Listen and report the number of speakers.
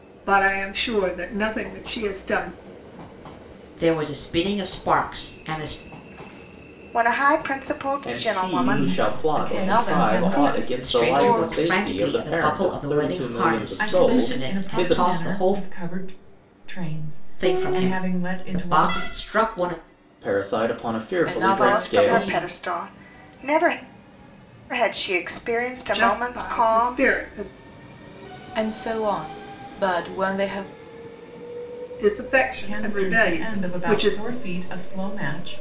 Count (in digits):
6